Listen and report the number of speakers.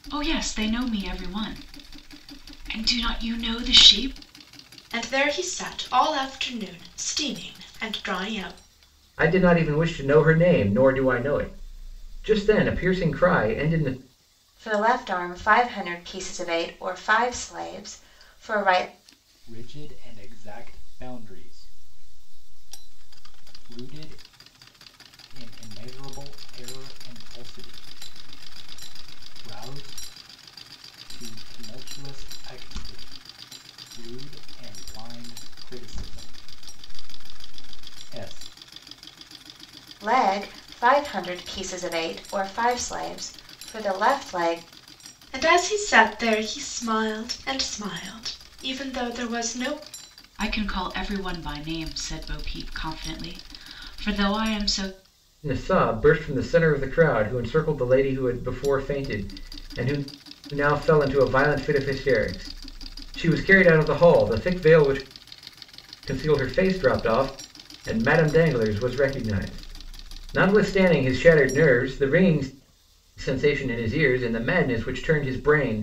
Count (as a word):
five